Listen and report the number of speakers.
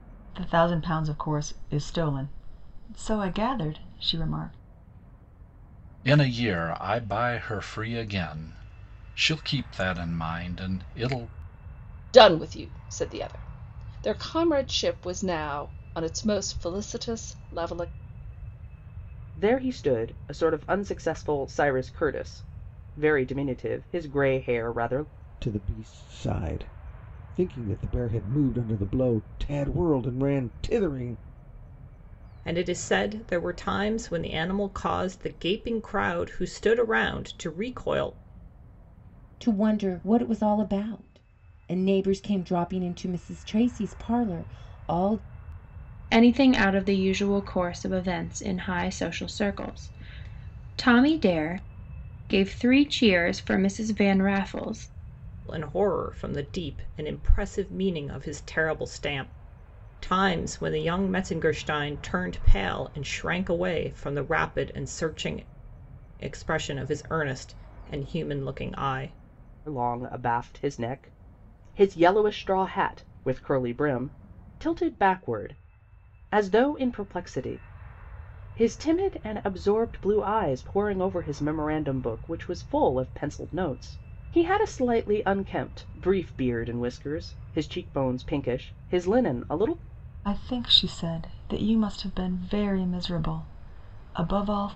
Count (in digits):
8